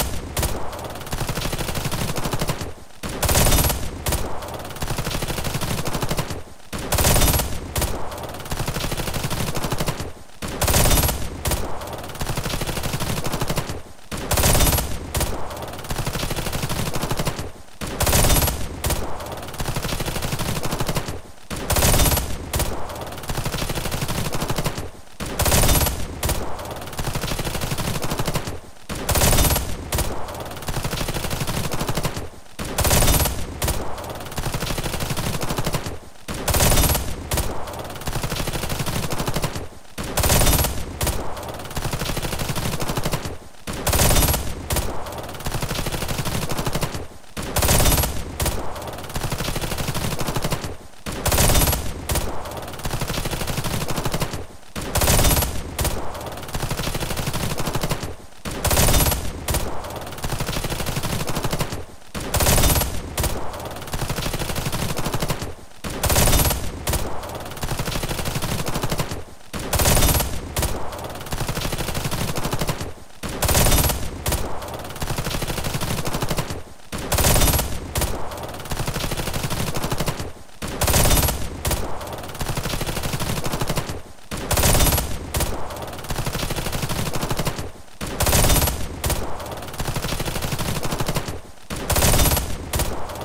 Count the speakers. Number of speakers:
zero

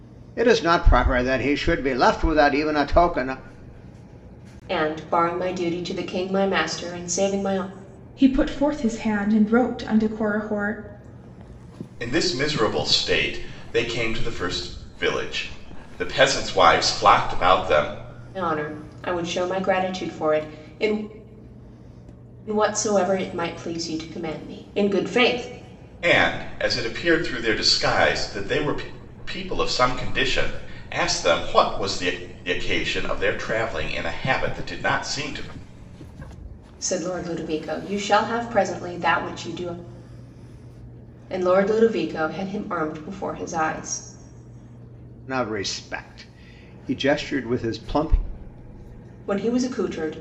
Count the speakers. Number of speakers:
four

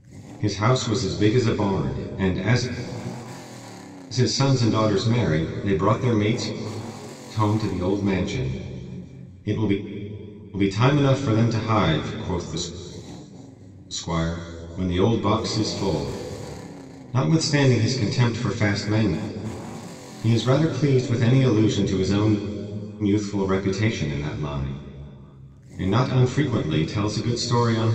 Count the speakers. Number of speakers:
one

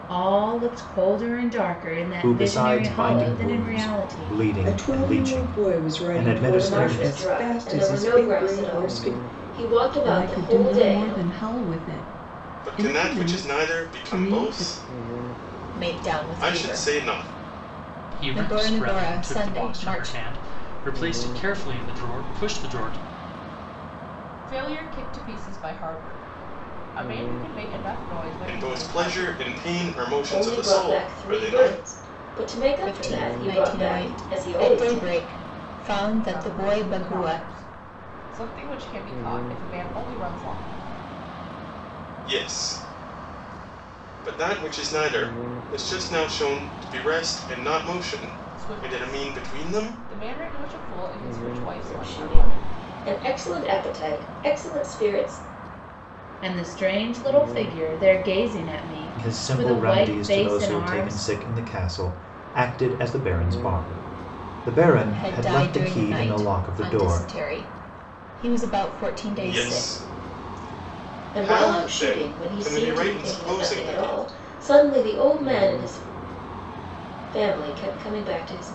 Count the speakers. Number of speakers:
nine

